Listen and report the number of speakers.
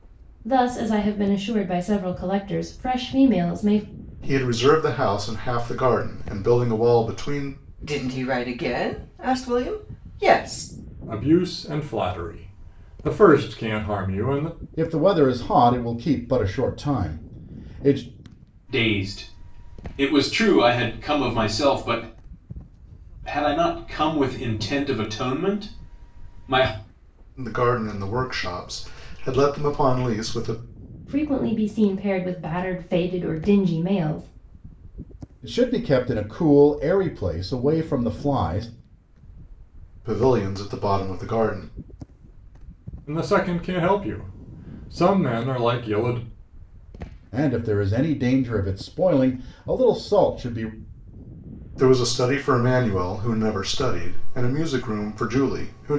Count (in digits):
6